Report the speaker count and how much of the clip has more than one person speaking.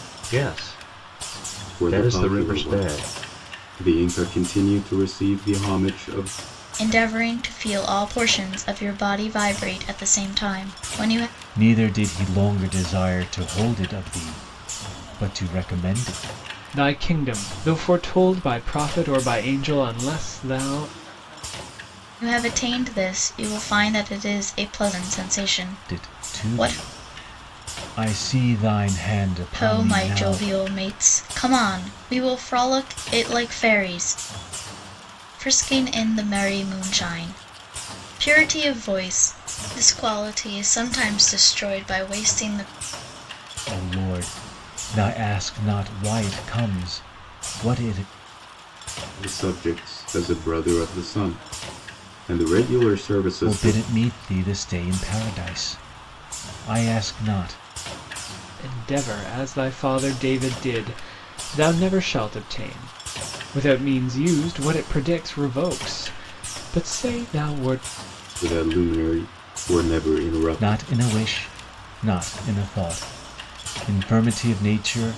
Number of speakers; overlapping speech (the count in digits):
5, about 5%